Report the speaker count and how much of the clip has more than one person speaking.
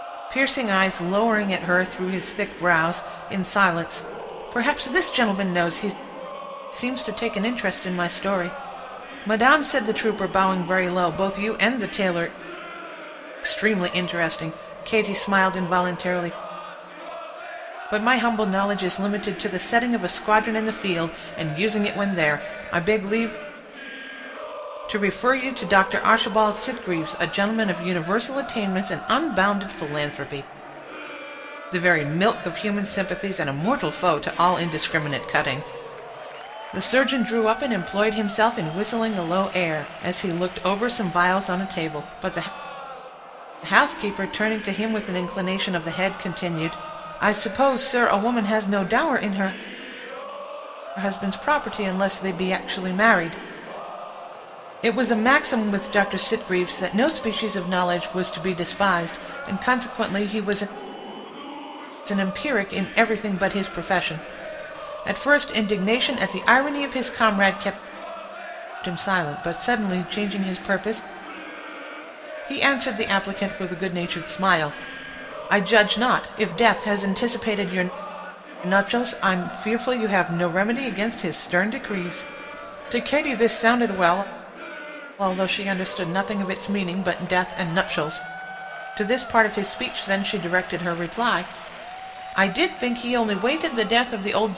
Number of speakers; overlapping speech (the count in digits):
1, no overlap